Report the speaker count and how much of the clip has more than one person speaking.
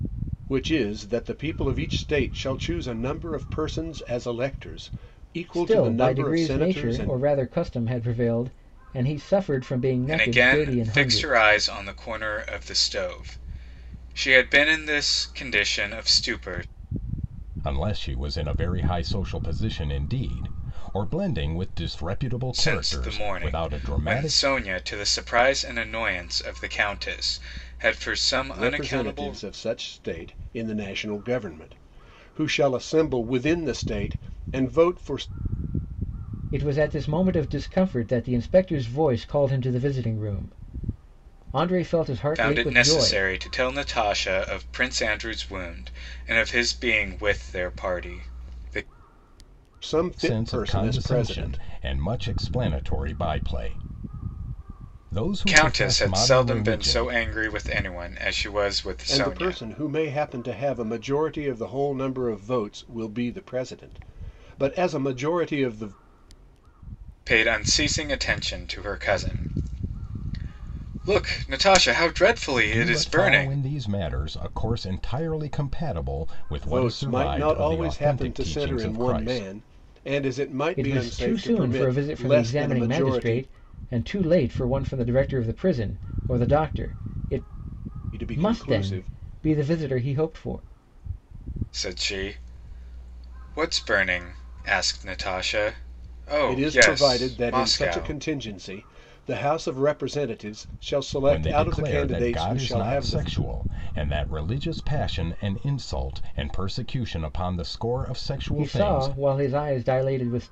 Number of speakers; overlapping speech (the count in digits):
4, about 20%